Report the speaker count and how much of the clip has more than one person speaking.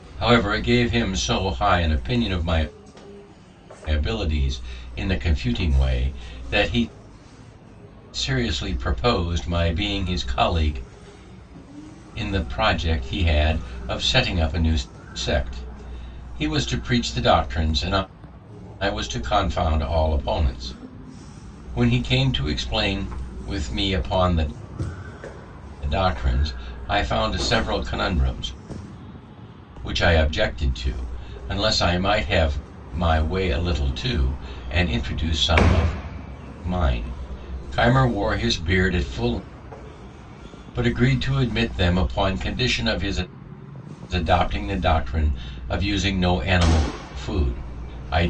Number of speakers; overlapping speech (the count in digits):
1, no overlap